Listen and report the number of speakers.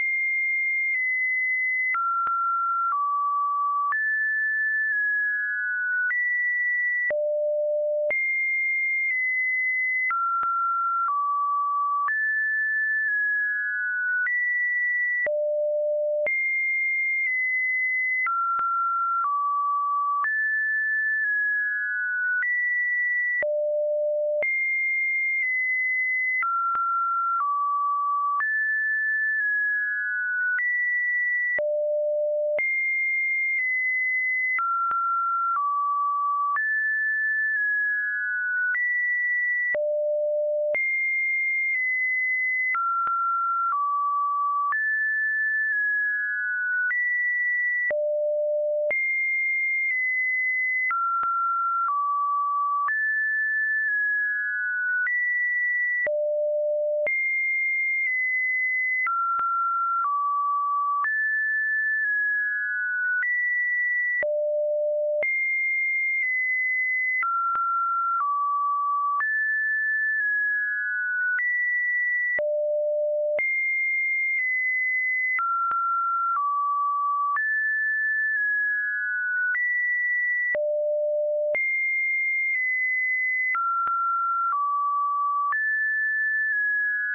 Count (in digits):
0